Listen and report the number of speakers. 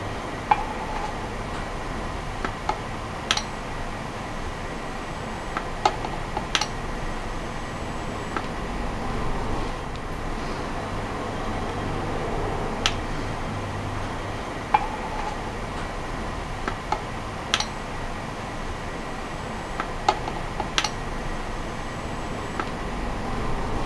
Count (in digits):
0